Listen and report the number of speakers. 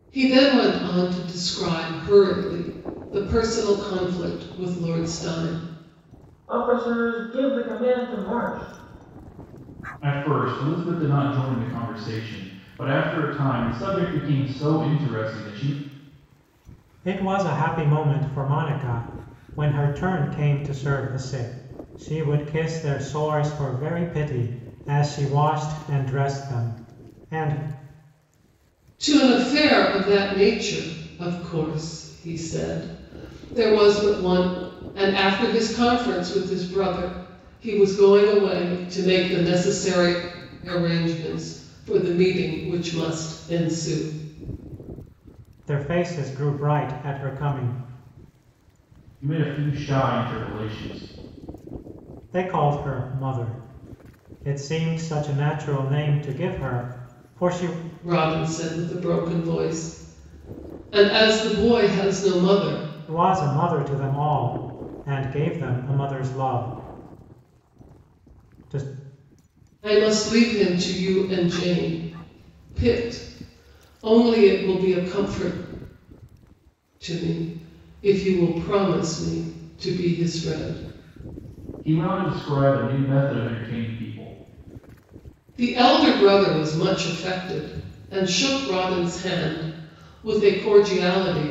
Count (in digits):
4